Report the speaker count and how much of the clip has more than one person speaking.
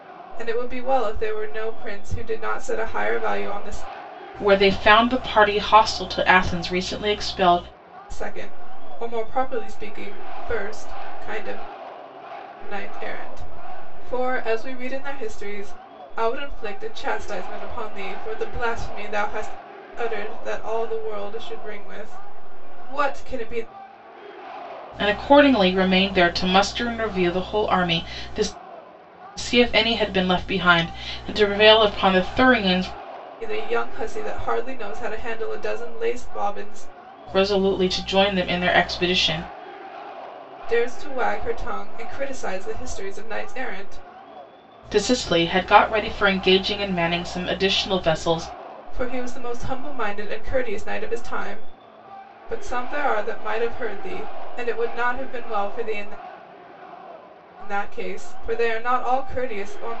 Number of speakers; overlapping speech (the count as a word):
two, no overlap